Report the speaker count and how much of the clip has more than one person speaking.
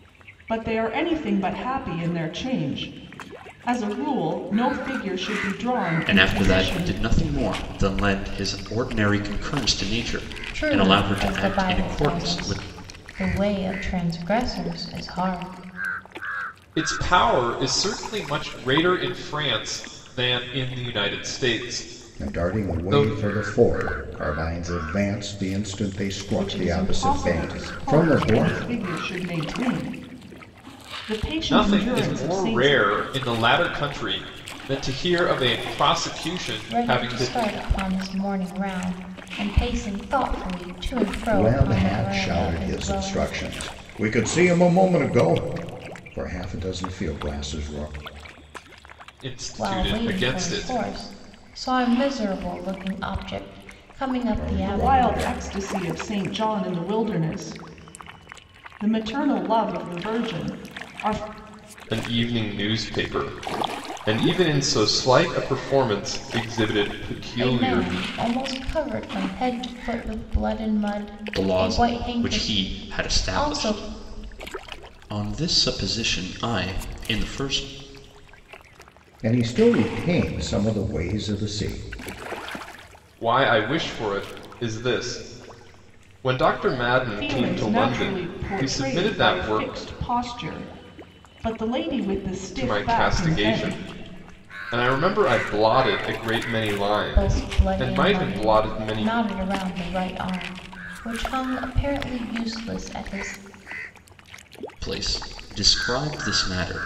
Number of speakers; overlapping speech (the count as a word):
five, about 20%